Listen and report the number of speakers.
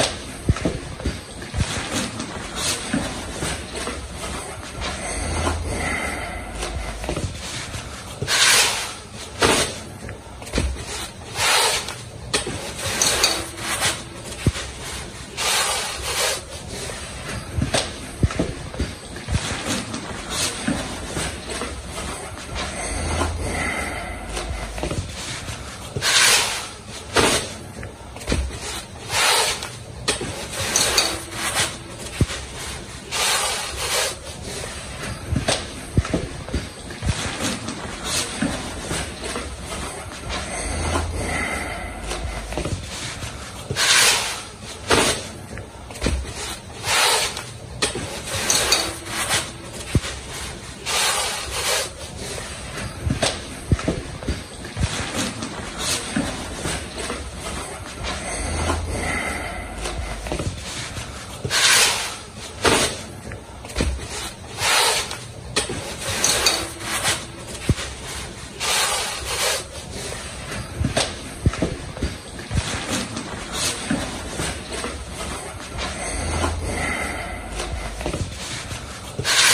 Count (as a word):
zero